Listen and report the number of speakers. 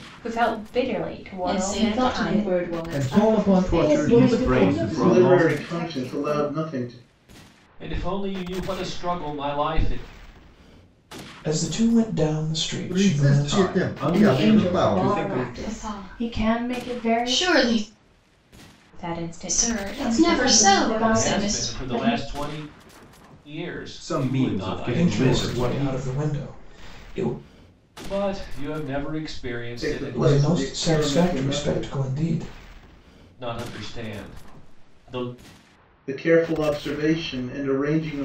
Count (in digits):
9